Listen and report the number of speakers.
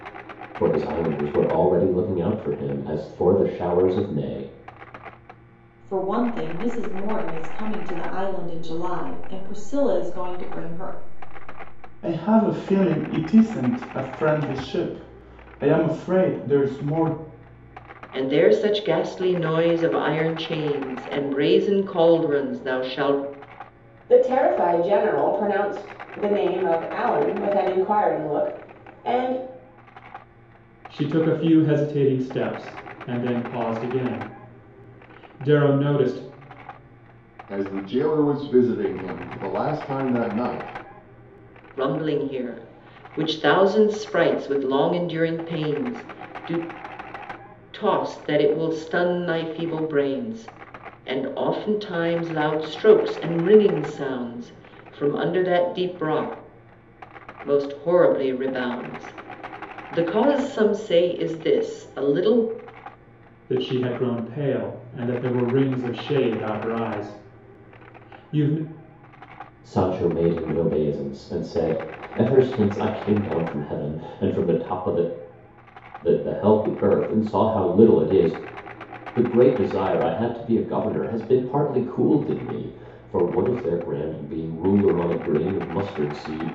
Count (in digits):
7